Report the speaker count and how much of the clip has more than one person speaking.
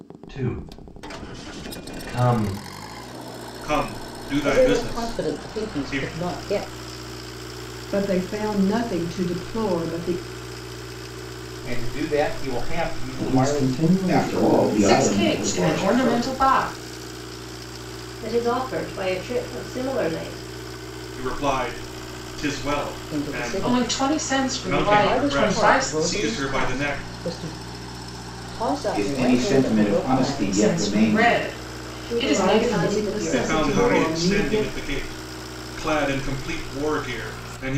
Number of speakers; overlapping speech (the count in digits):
9, about 37%